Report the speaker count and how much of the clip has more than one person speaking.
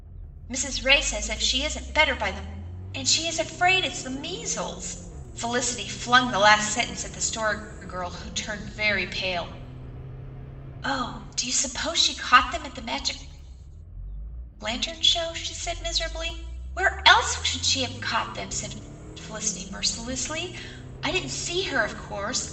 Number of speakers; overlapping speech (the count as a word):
one, no overlap